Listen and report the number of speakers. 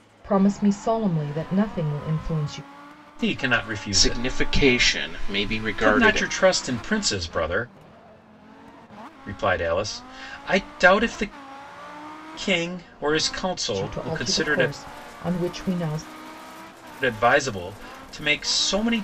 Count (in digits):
3